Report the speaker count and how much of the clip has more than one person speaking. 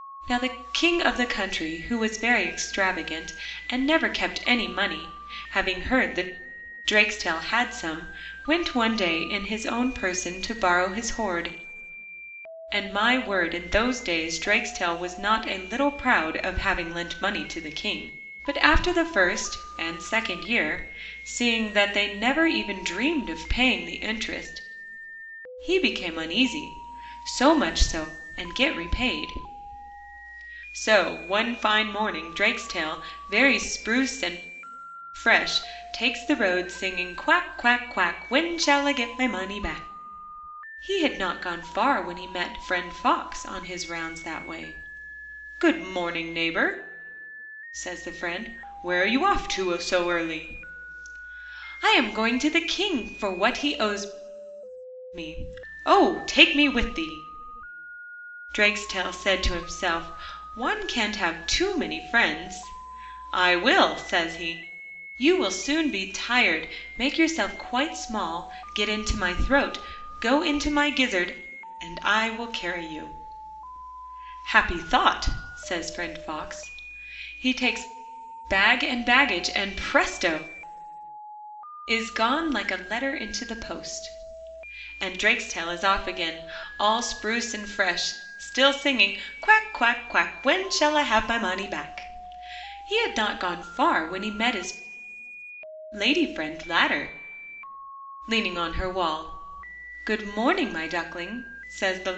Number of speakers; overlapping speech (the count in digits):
1, no overlap